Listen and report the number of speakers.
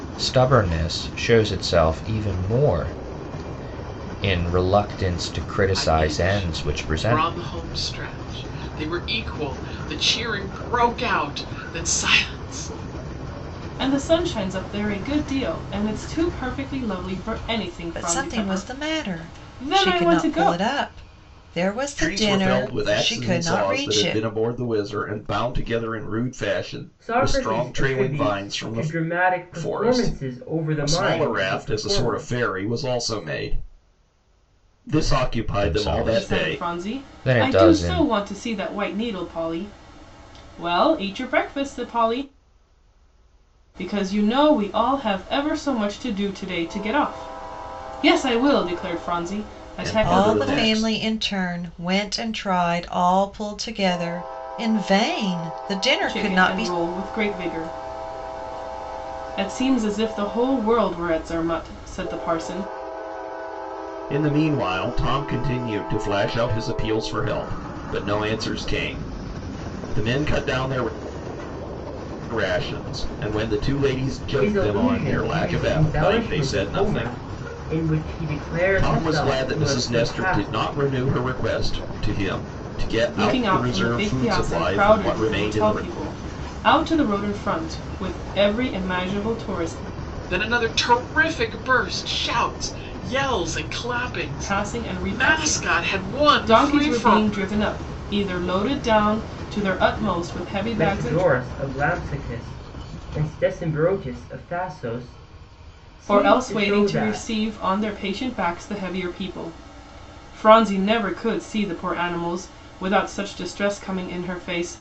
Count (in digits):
6